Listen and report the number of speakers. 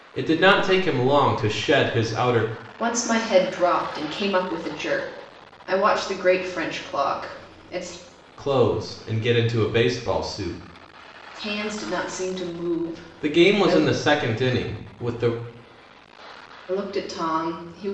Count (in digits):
2